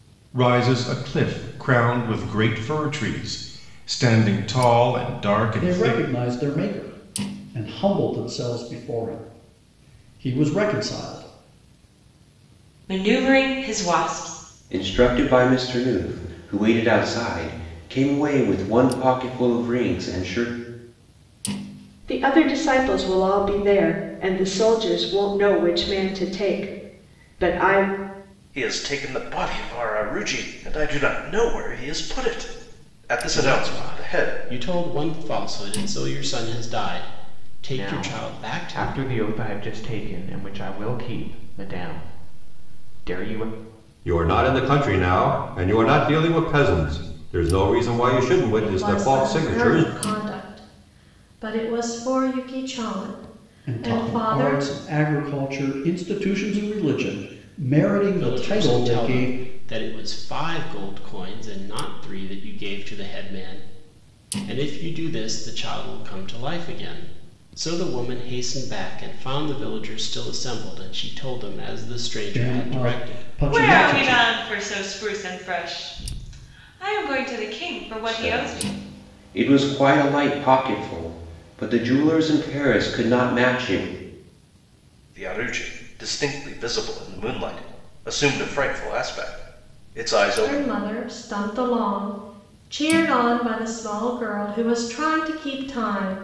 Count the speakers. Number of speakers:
10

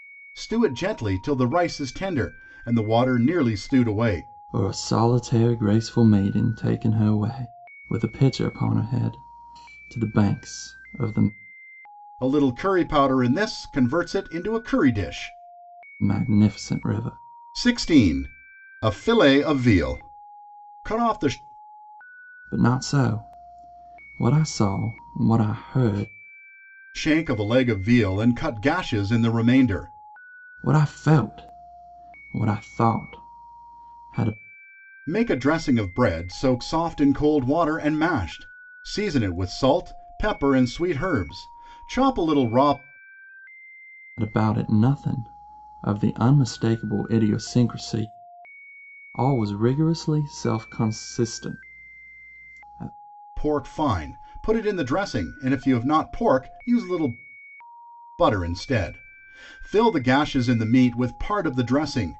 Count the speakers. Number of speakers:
2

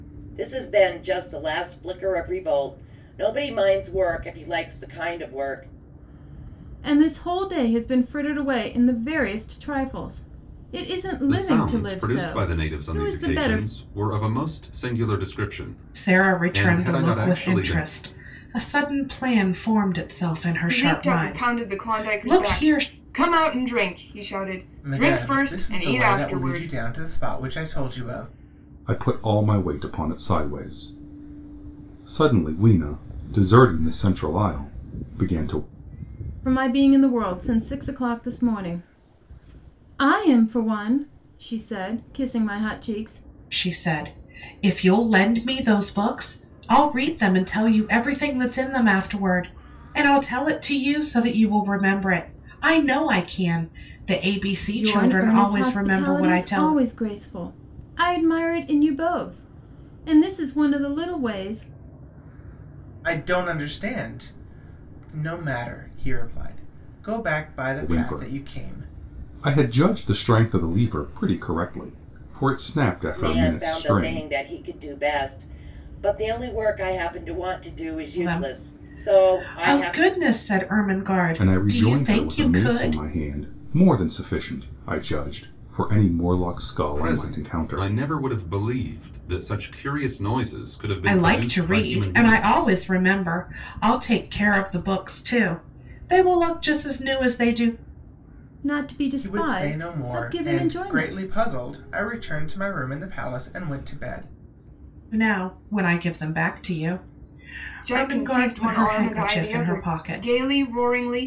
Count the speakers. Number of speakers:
7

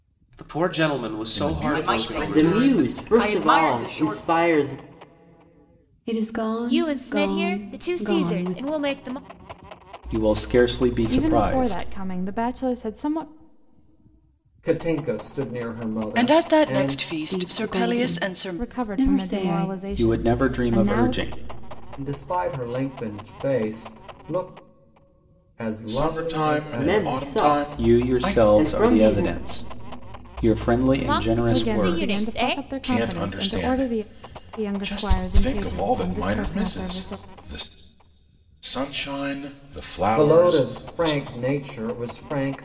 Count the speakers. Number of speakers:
10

